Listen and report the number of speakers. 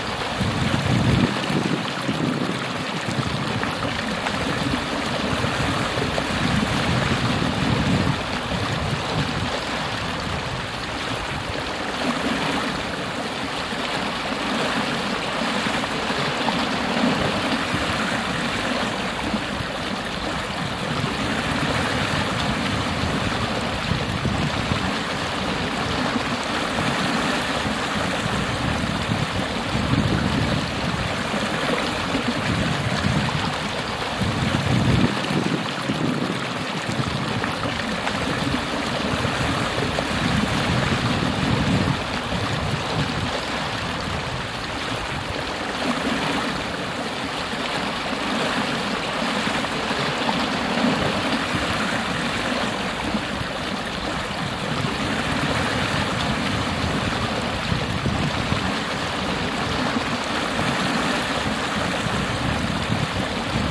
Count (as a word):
zero